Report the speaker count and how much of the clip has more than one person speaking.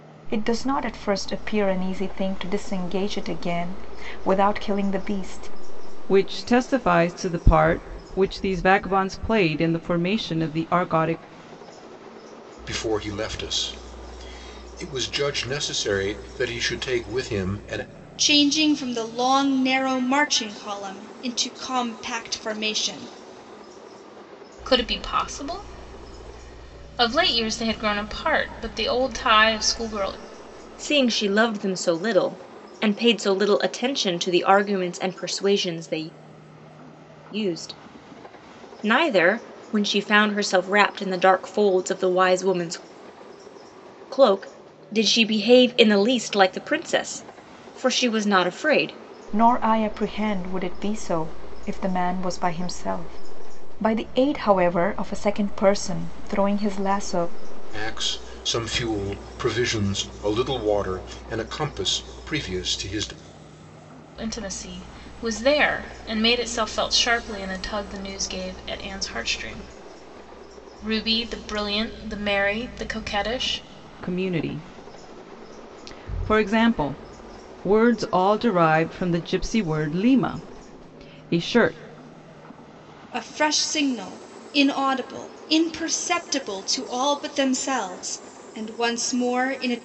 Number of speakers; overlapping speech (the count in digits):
6, no overlap